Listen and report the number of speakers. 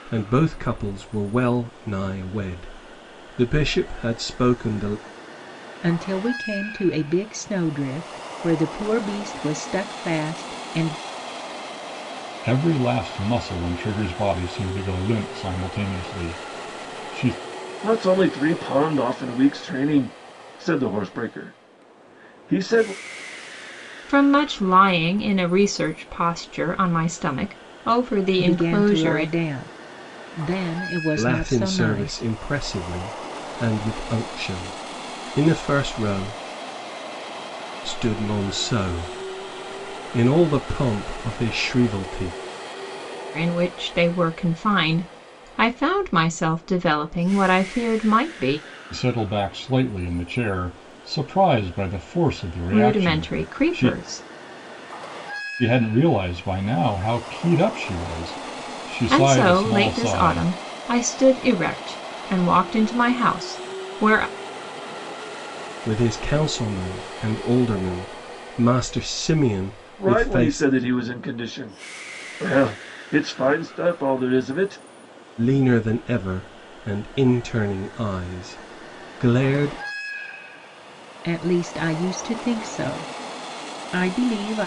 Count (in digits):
5